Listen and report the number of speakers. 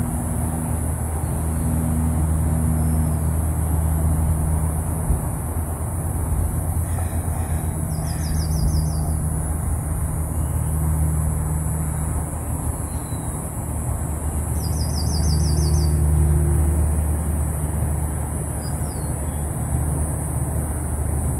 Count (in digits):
0